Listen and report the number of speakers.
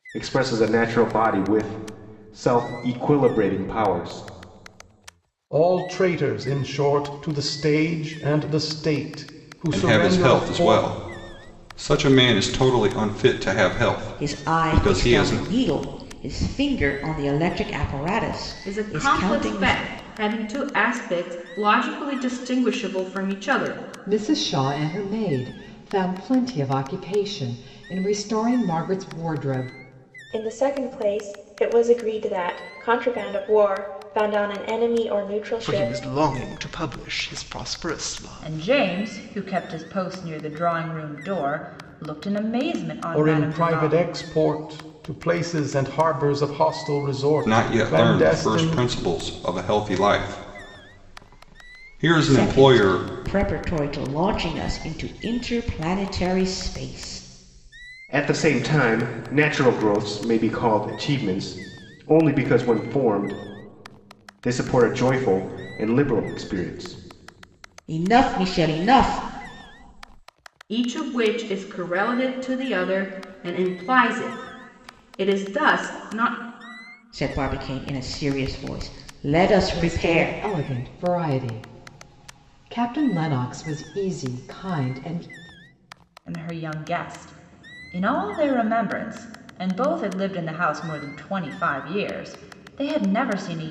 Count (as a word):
nine